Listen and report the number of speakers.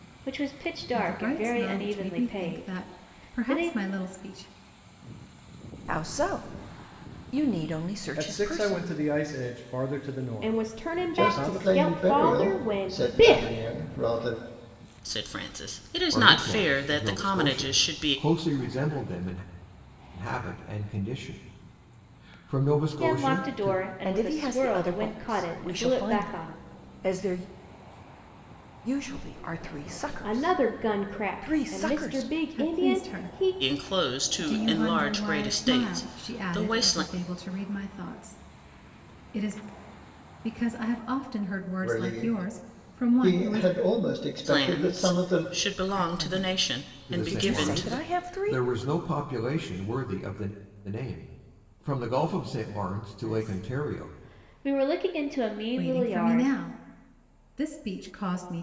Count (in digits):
8